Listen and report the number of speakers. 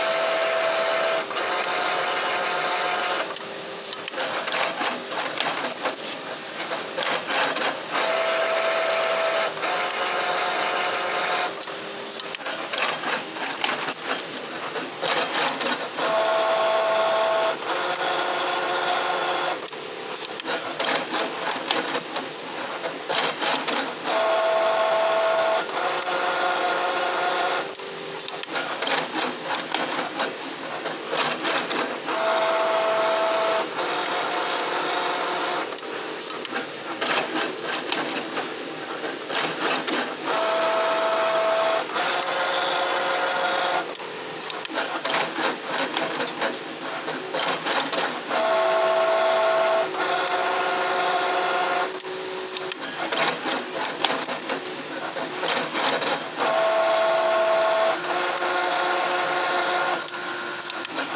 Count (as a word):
zero